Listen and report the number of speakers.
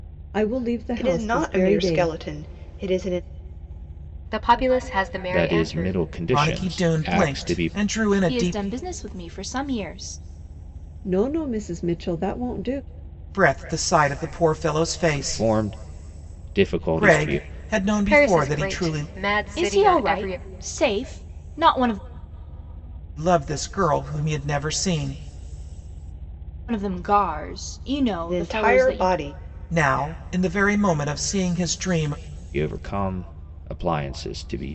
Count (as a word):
six